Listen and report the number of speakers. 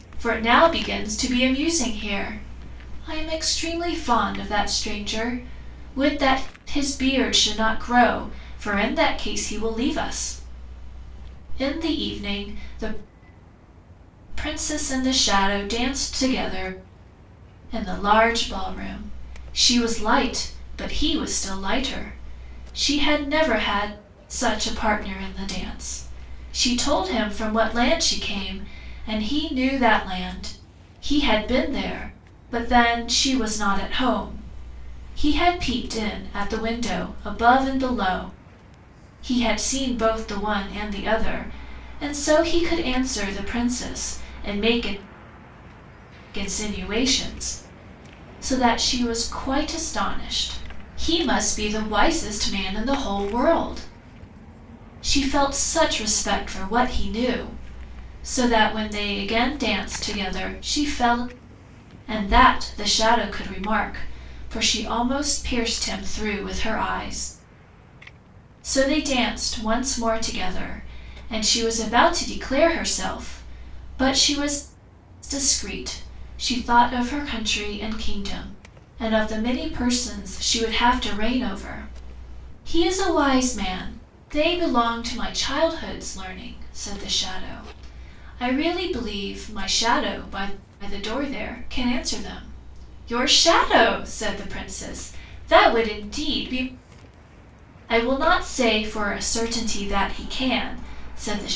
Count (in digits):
1